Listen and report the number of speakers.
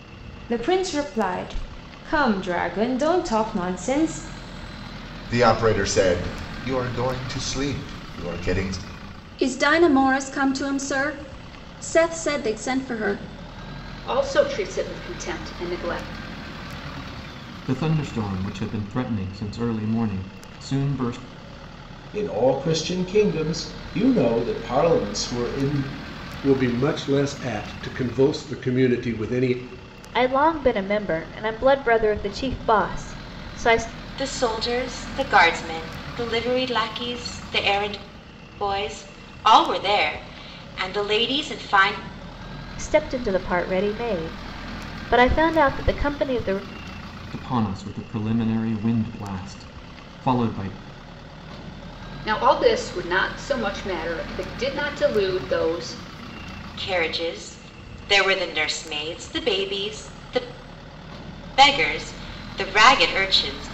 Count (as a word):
nine